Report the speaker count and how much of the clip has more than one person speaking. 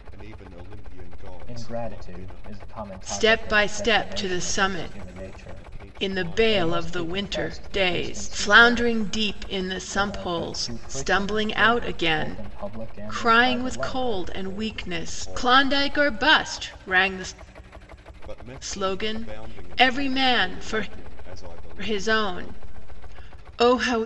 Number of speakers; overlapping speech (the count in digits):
3, about 60%